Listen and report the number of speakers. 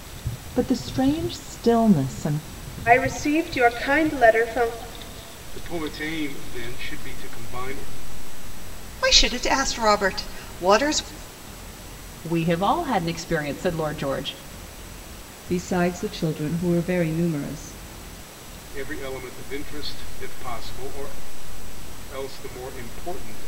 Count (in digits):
6